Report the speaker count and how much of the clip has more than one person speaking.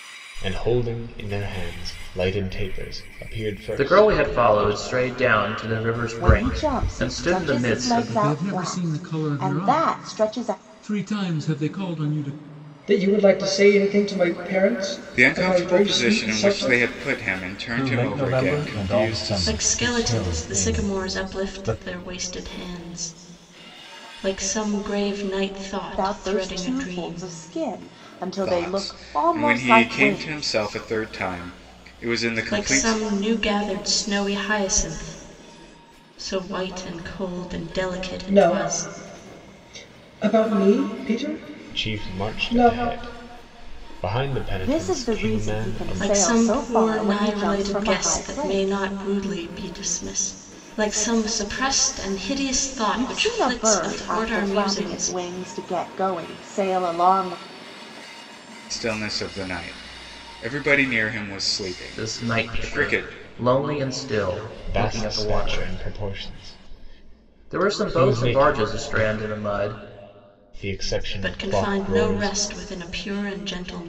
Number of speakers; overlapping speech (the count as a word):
eight, about 39%